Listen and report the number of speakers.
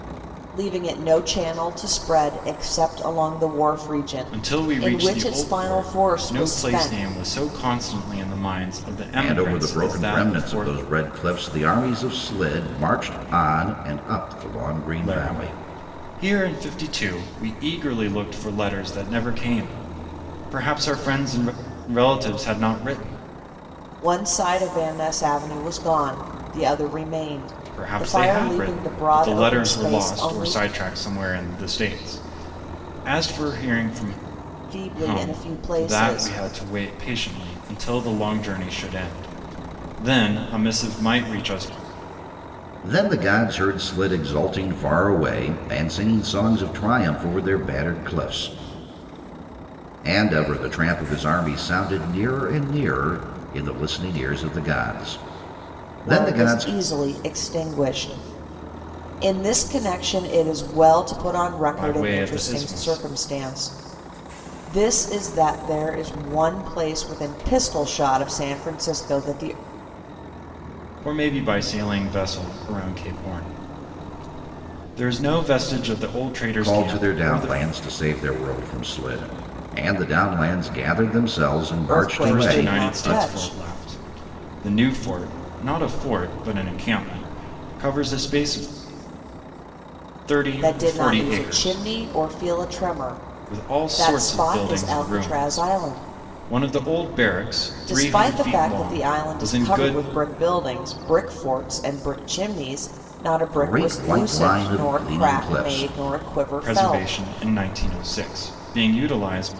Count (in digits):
3